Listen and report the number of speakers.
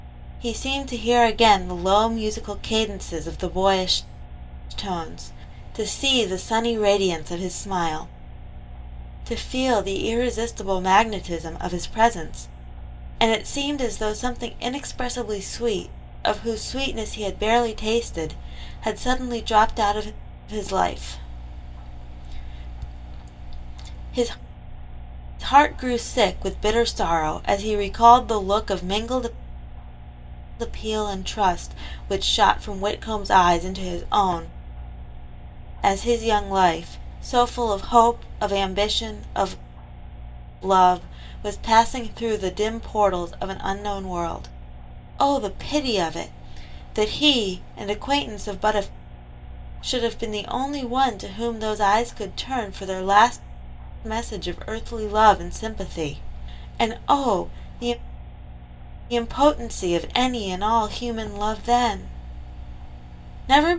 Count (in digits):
1